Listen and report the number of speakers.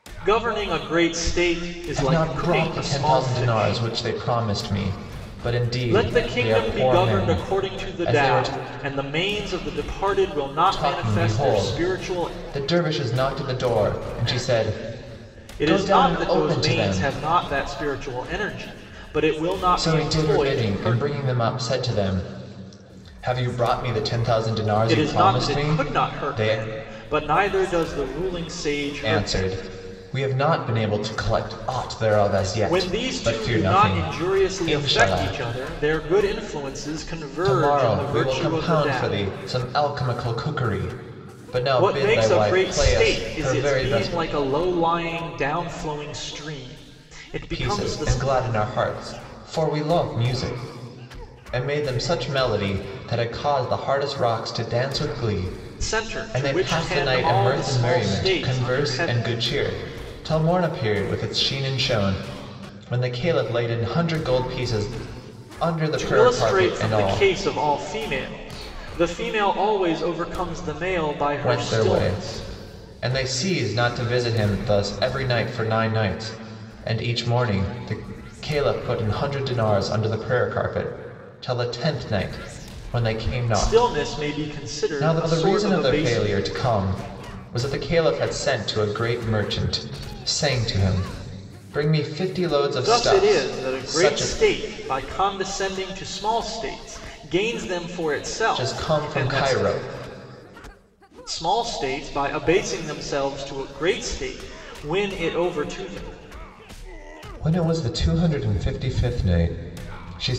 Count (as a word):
two